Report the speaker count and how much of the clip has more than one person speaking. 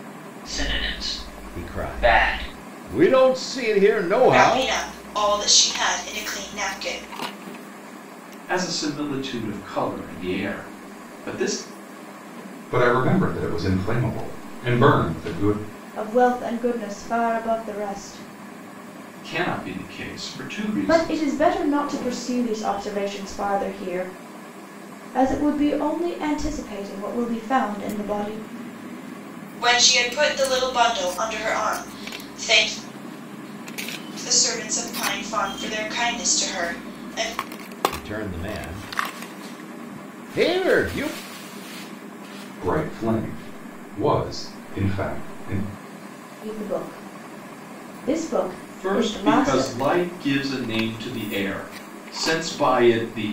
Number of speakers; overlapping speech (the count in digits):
6, about 5%